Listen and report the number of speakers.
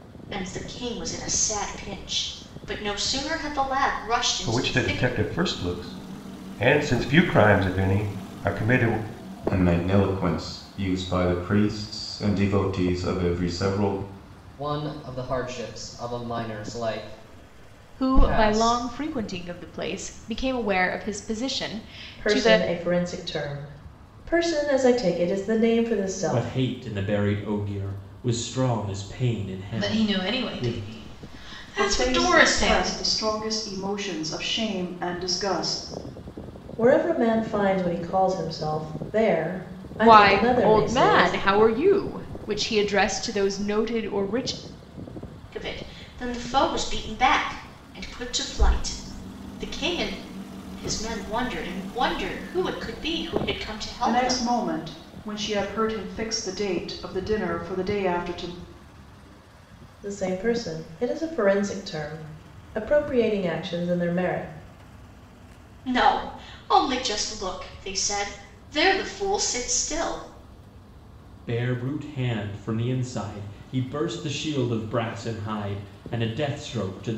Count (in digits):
9